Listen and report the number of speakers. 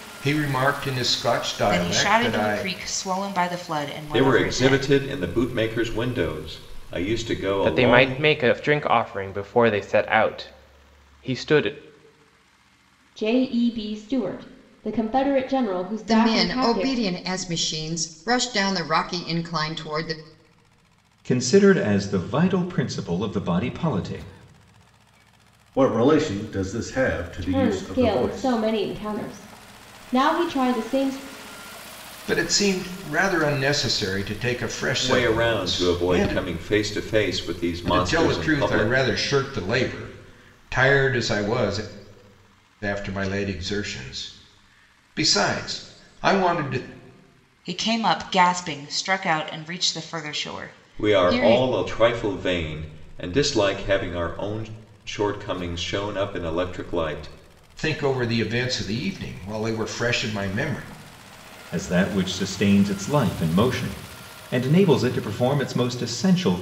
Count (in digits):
8